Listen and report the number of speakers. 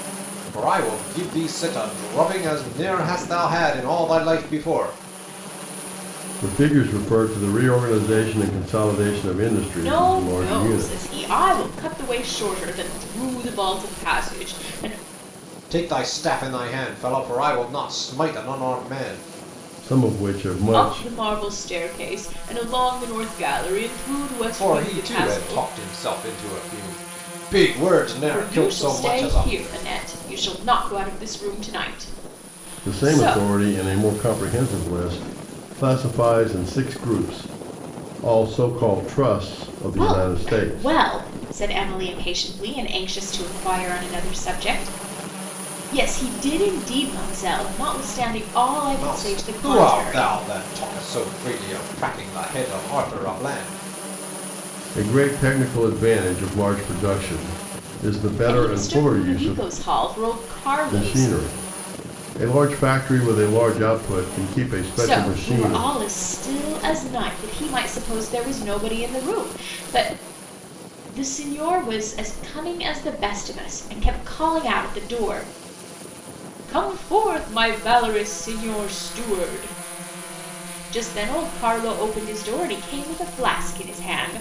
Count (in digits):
3